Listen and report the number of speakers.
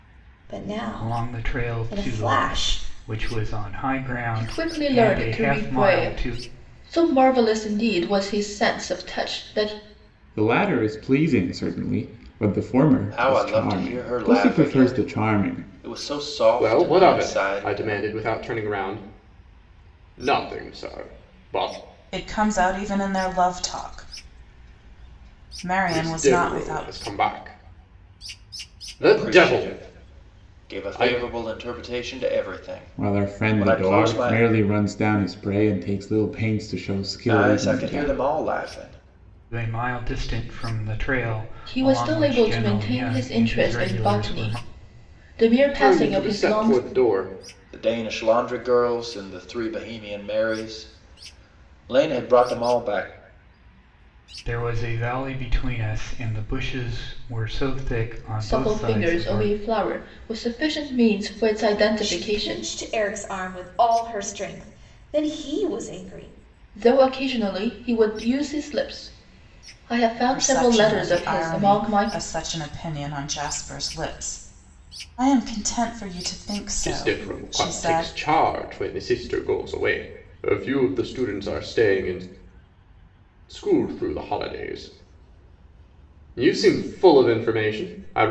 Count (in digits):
7